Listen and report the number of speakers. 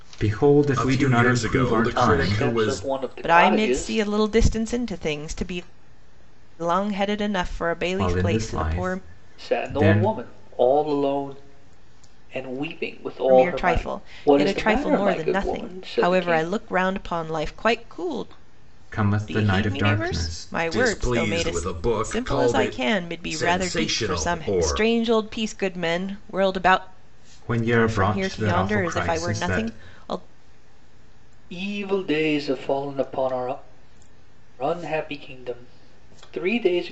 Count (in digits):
4